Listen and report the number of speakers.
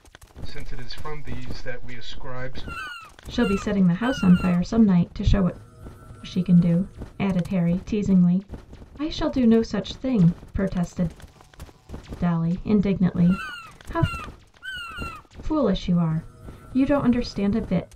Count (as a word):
two